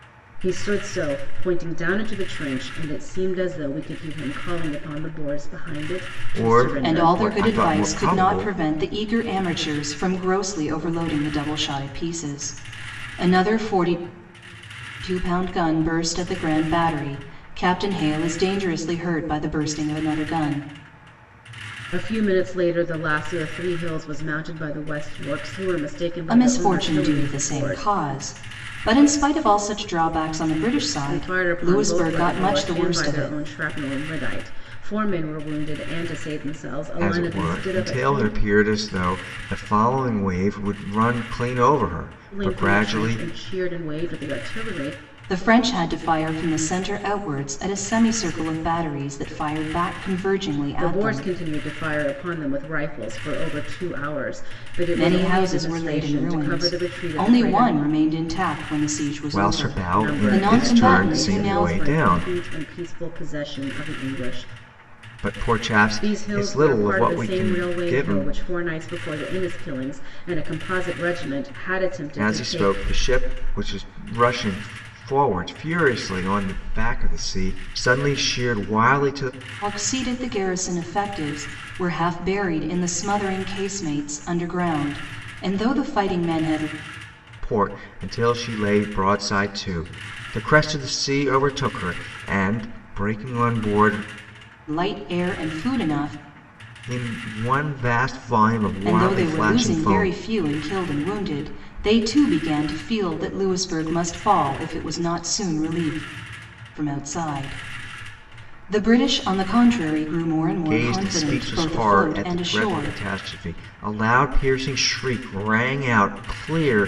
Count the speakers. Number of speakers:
3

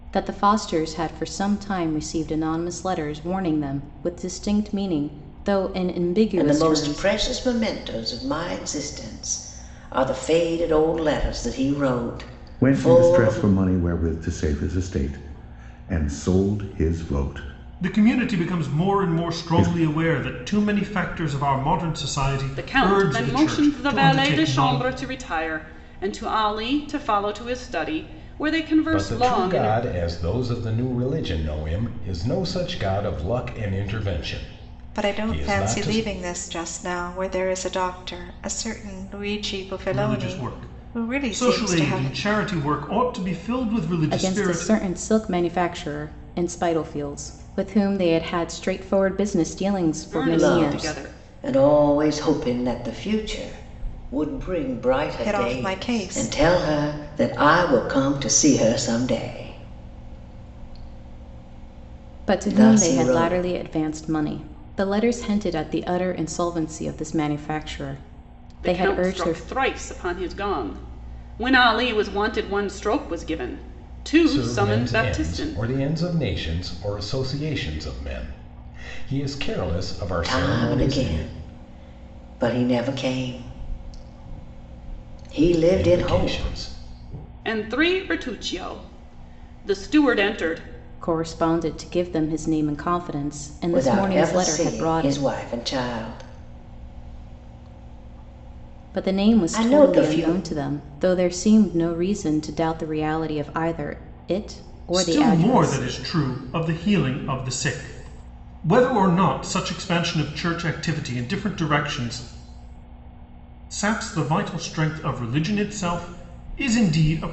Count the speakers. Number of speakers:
7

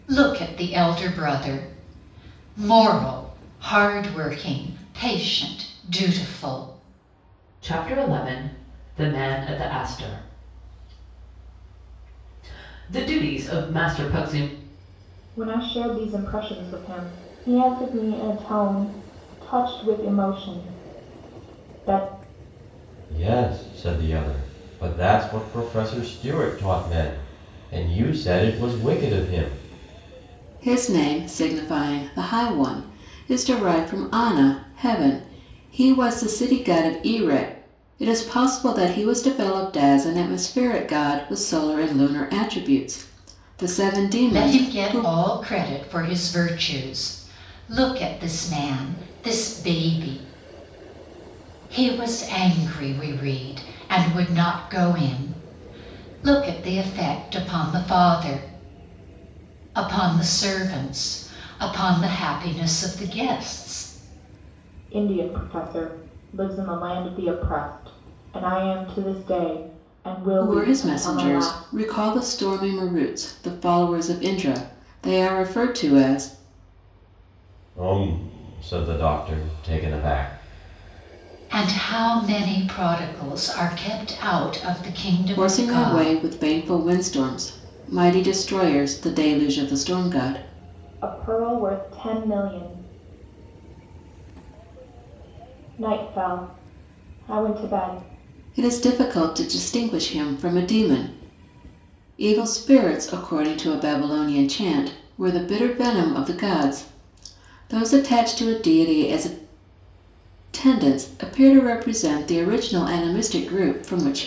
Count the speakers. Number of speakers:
5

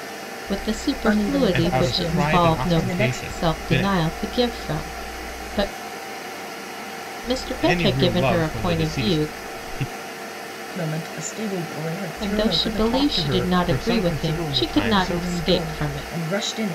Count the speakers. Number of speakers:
3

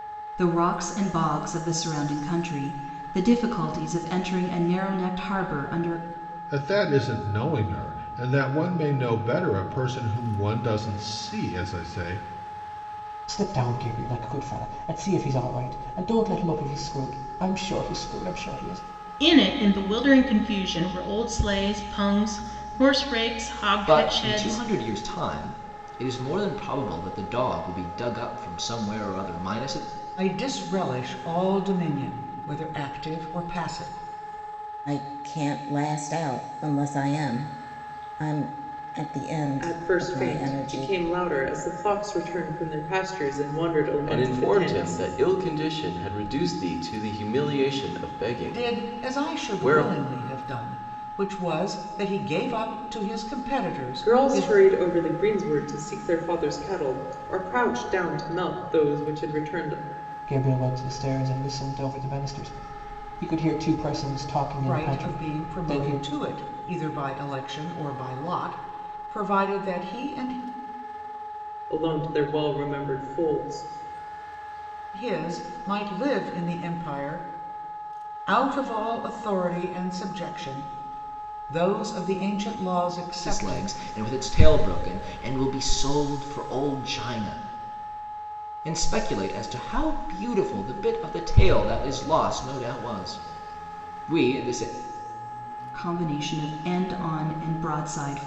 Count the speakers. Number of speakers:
9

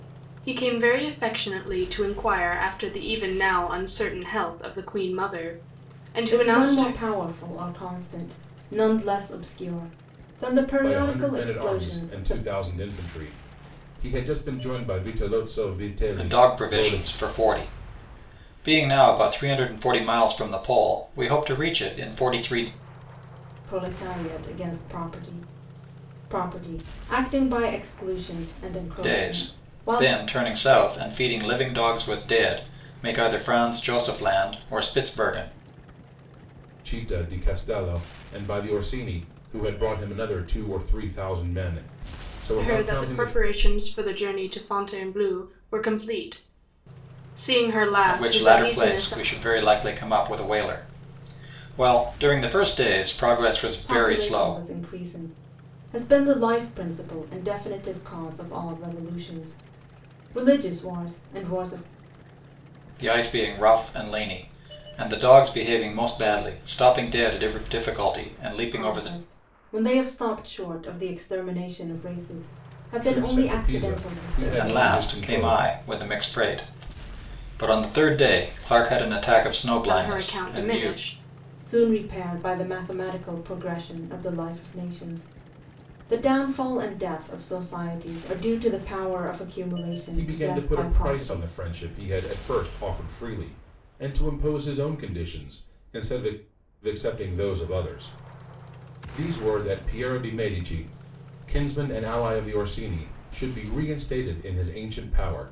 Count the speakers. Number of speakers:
4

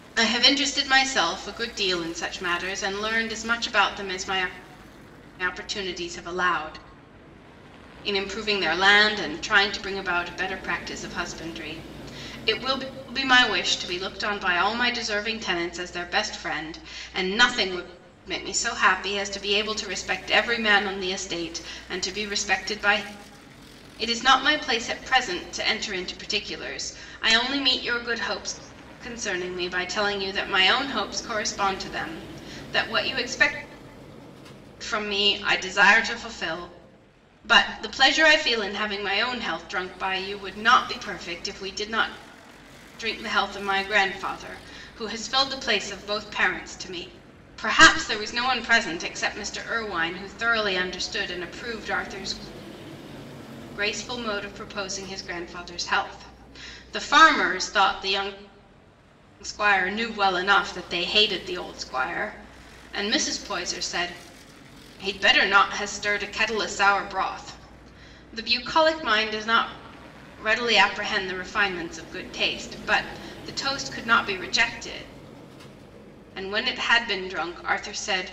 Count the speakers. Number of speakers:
1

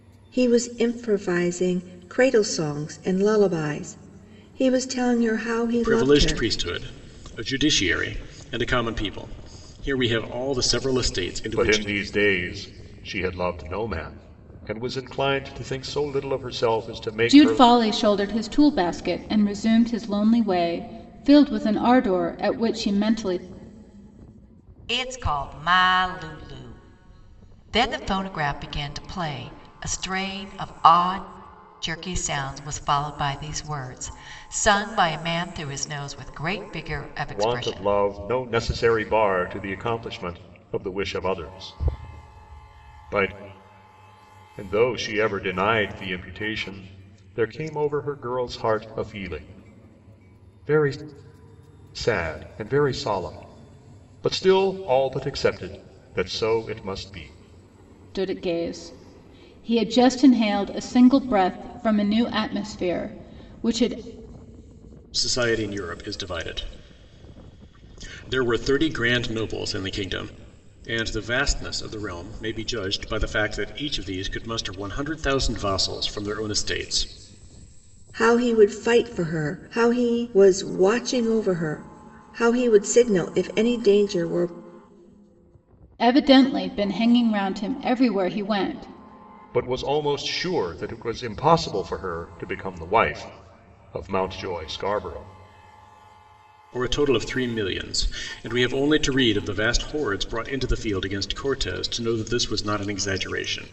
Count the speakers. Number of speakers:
5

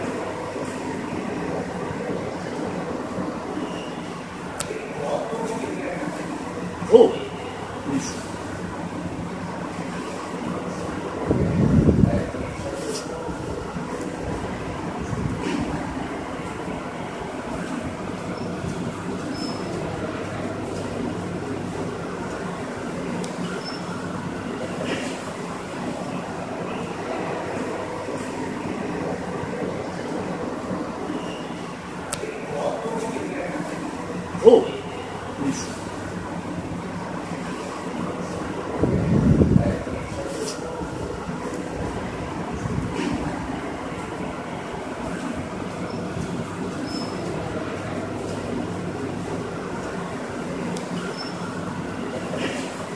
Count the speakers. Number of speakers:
0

